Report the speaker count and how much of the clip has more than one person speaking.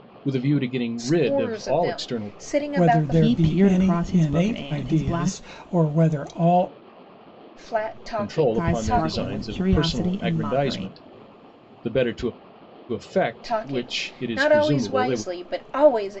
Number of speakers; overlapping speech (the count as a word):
four, about 55%